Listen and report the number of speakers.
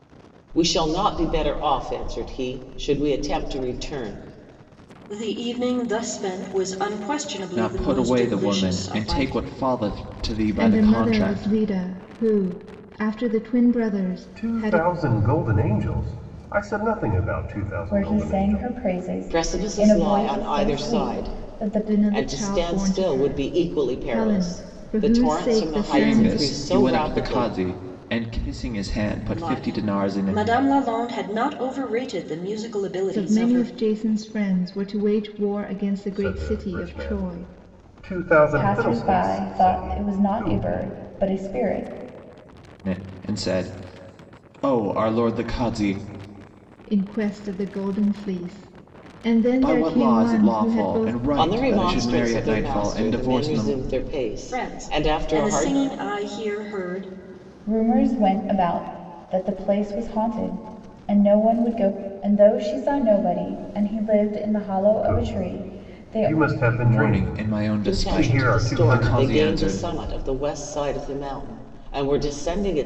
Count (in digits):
6